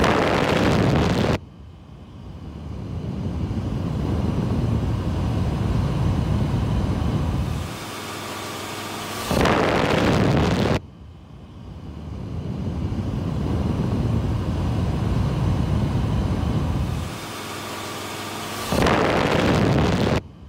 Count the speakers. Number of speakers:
0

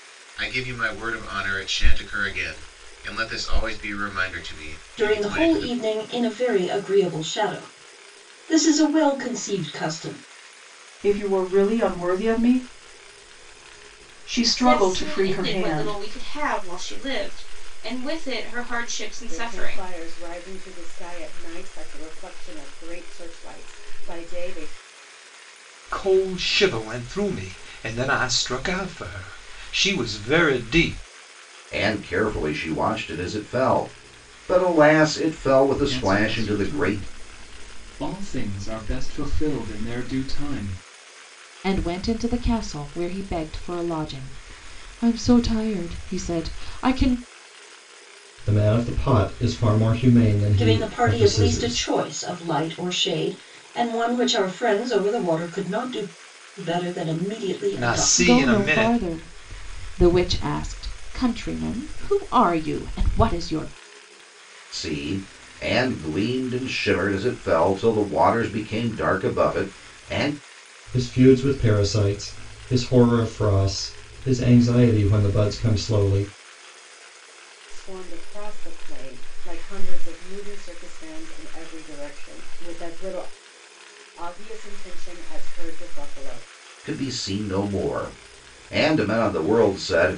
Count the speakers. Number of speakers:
10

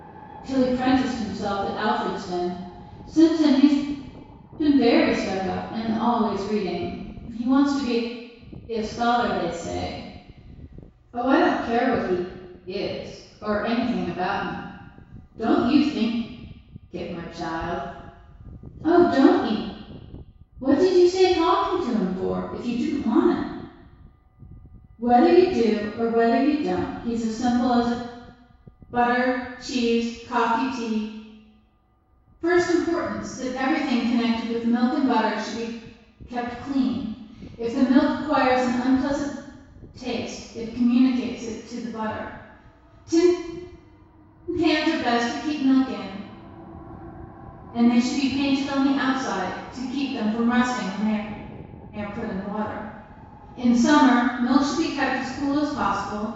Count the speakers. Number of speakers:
1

